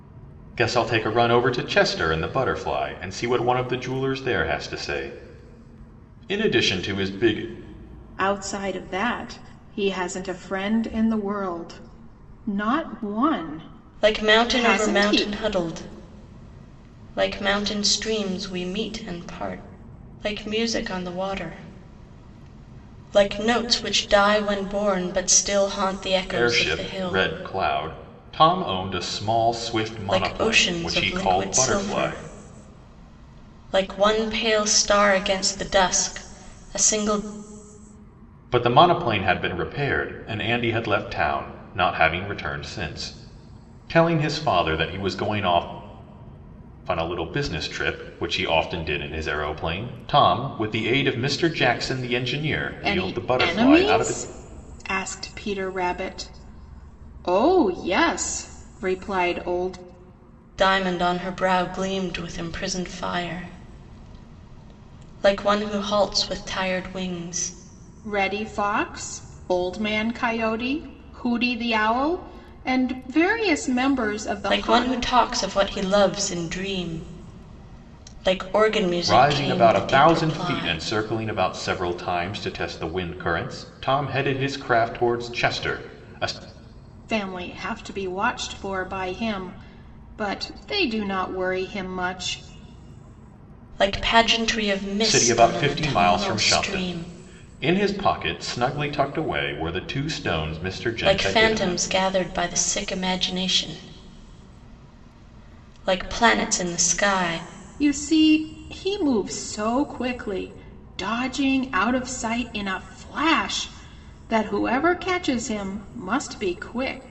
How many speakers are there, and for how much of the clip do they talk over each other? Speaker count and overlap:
3, about 10%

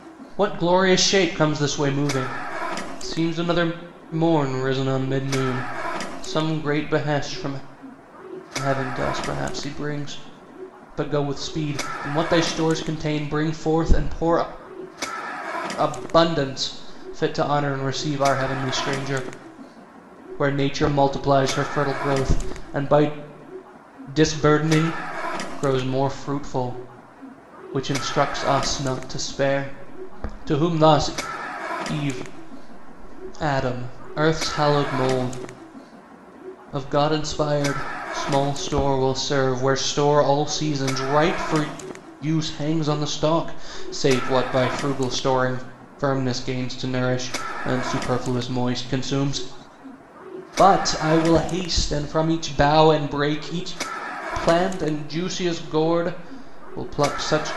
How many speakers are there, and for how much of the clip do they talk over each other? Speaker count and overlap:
1, no overlap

